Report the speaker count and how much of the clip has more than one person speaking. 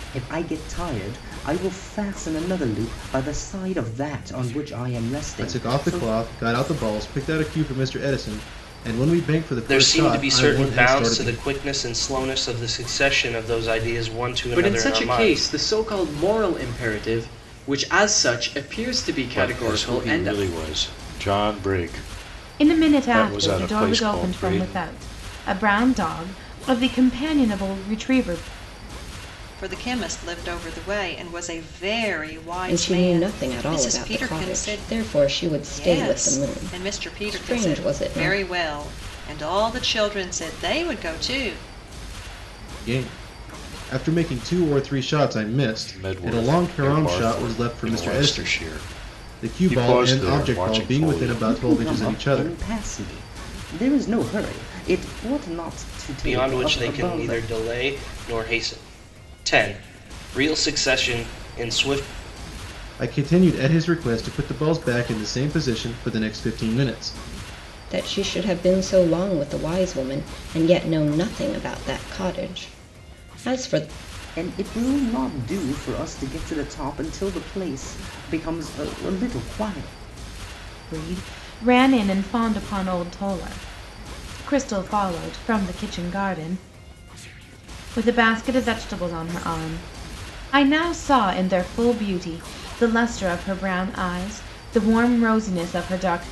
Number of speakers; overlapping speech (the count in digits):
8, about 20%